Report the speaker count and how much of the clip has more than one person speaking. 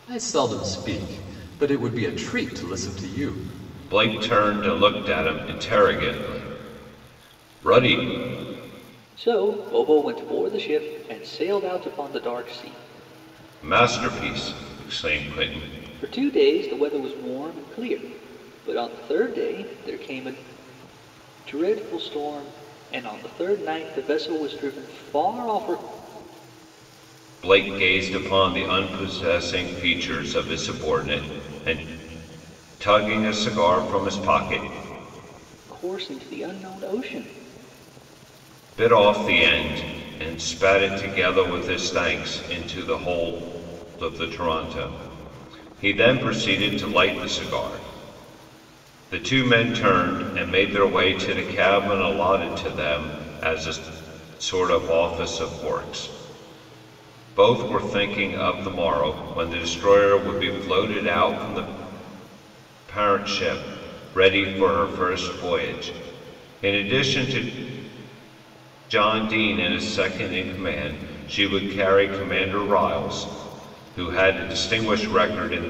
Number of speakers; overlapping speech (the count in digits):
3, no overlap